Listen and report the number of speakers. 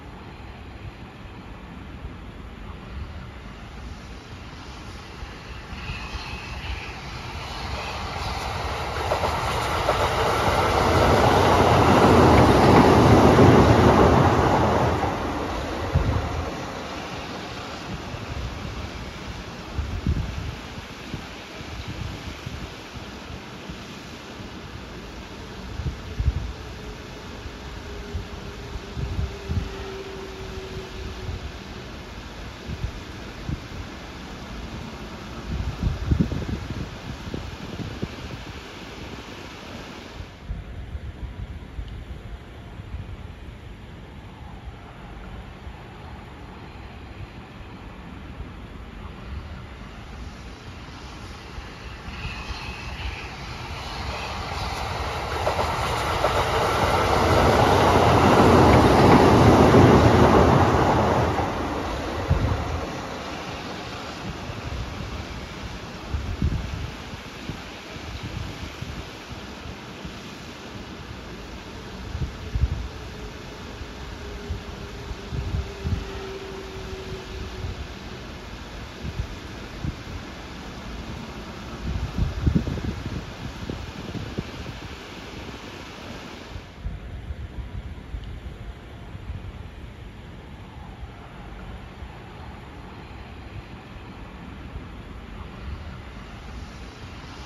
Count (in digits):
0